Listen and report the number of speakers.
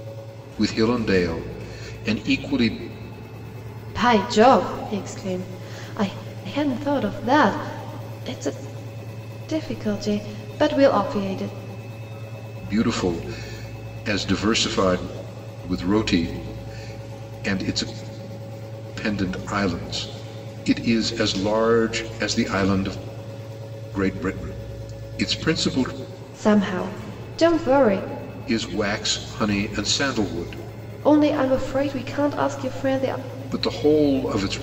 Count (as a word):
two